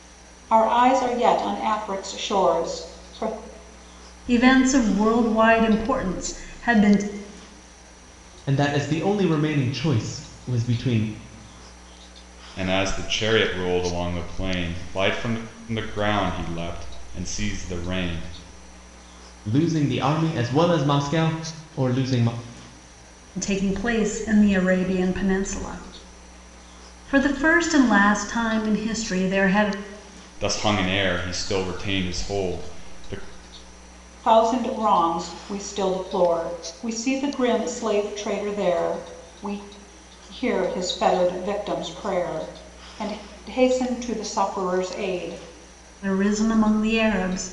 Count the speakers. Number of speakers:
four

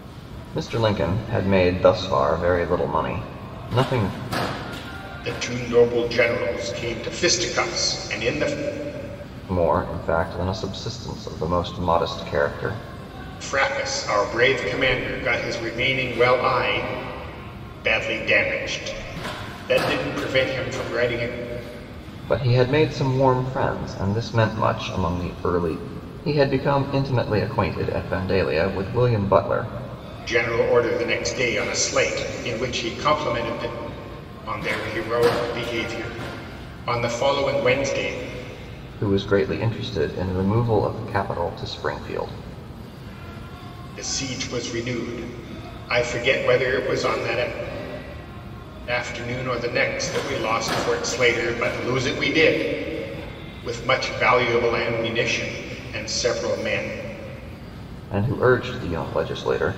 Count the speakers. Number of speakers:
two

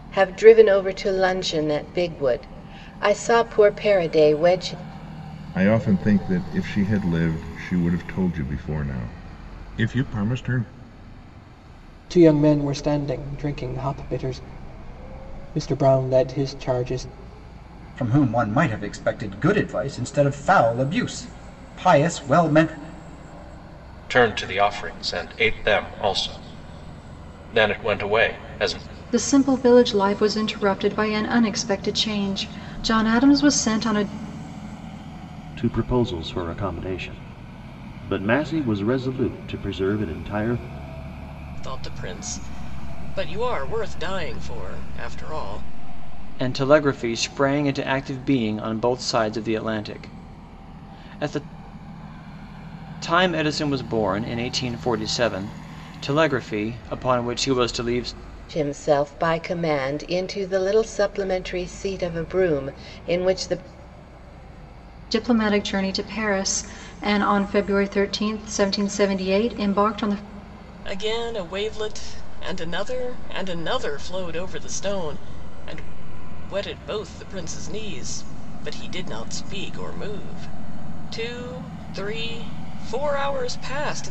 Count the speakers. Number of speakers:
nine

